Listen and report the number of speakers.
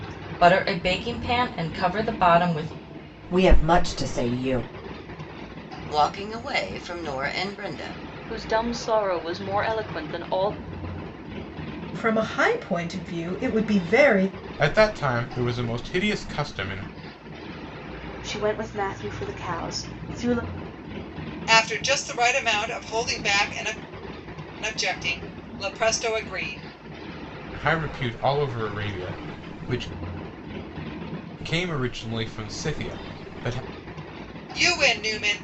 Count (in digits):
8